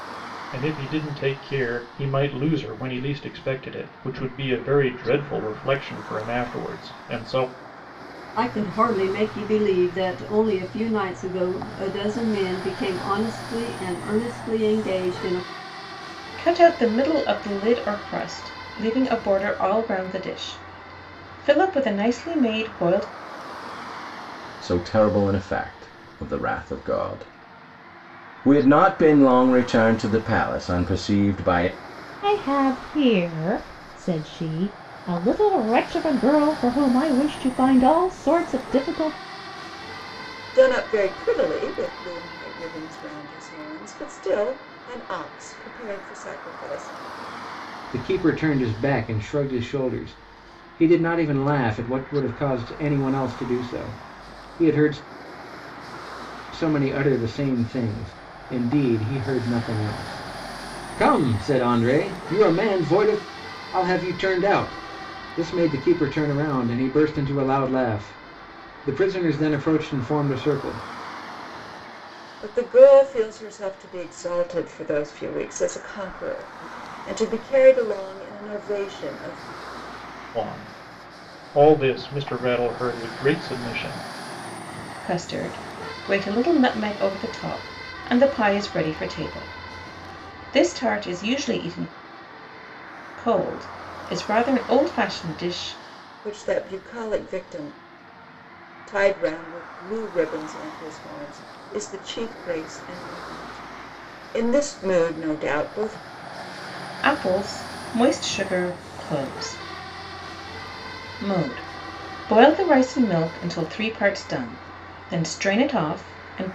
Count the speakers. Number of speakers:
seven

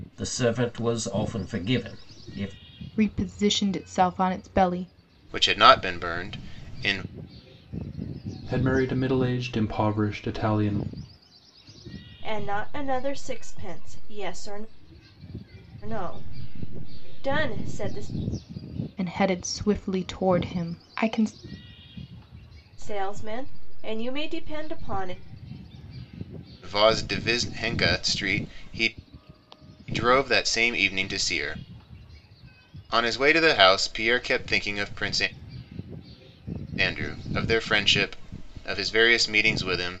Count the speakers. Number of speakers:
five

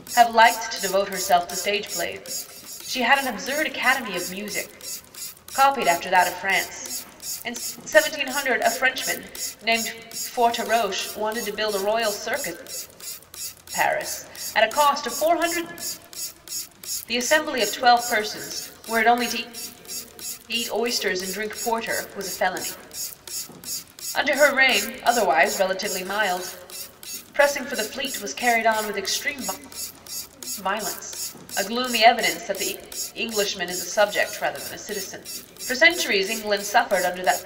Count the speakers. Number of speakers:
one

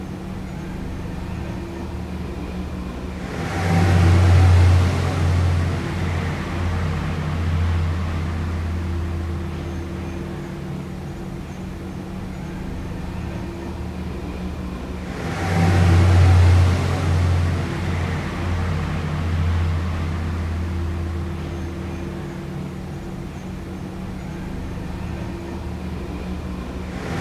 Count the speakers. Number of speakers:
zero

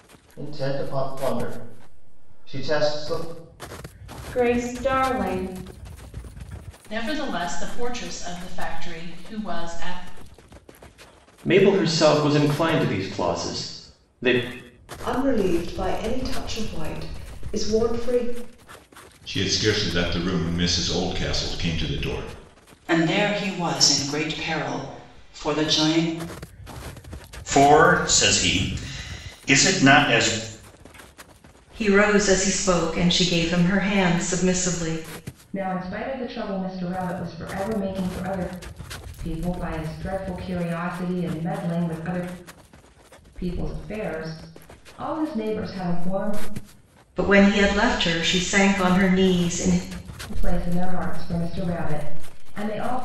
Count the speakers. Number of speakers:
ten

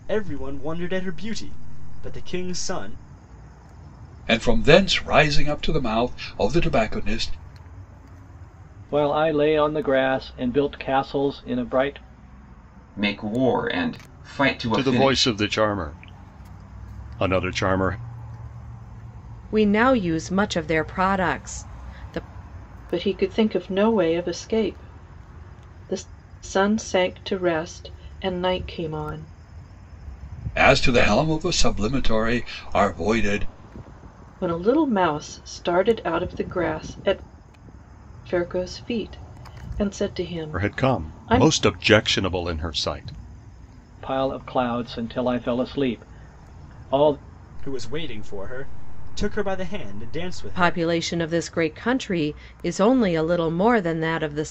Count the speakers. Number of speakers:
seven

